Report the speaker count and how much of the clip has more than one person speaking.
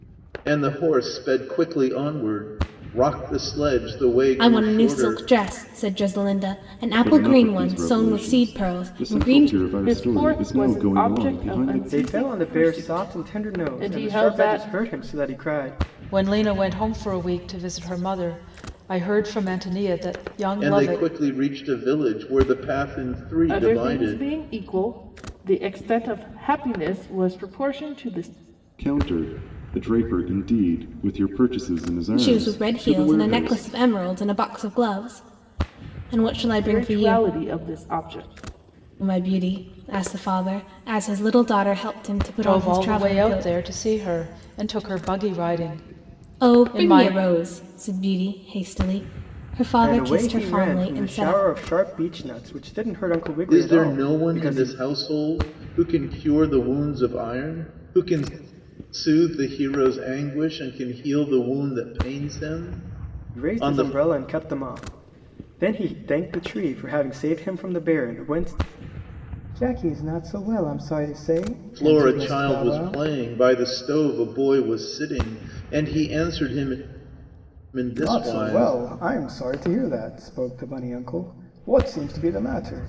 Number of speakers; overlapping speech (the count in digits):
6, about 24%